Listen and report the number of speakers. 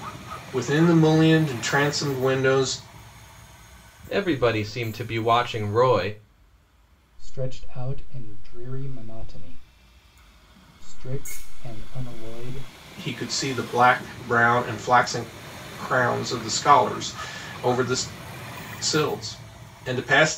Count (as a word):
three